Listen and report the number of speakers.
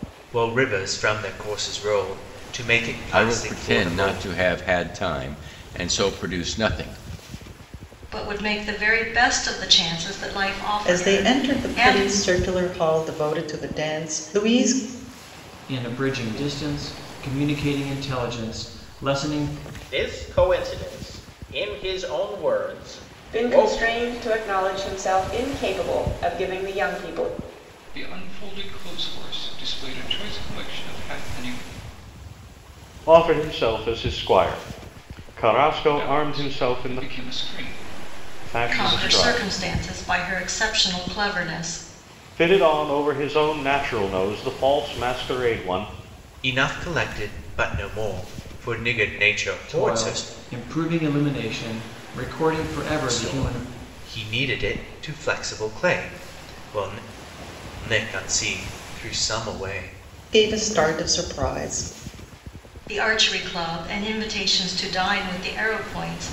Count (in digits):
9